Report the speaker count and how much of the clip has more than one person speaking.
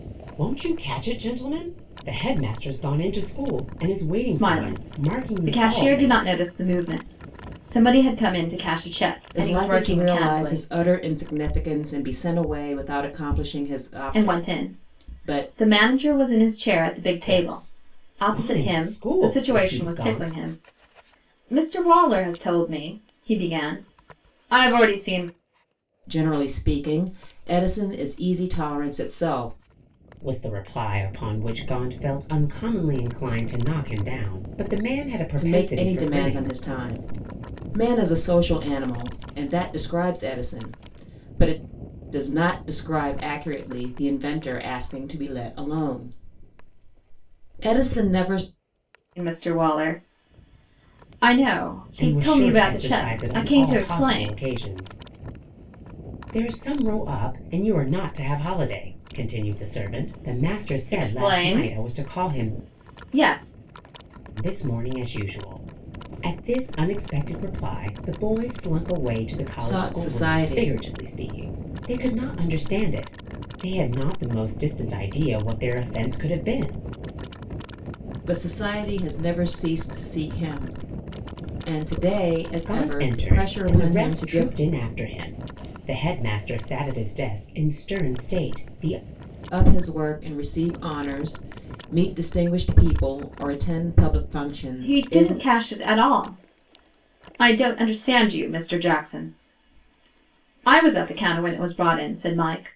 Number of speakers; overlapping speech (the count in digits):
3, about 17%